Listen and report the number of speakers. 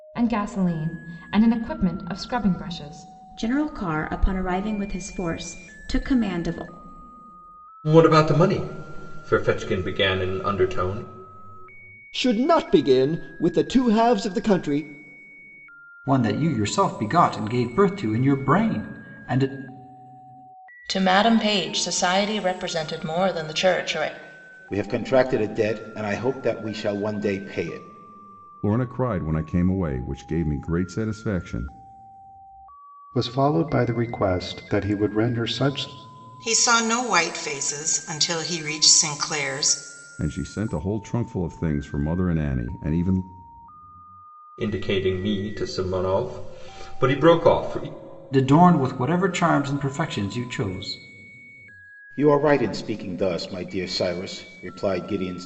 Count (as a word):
ten